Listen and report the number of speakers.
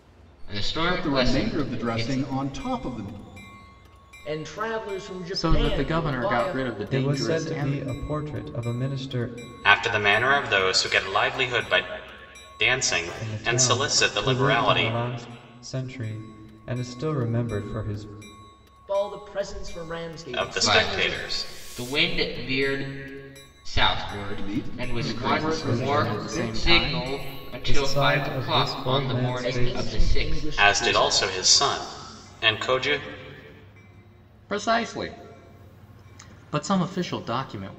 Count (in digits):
6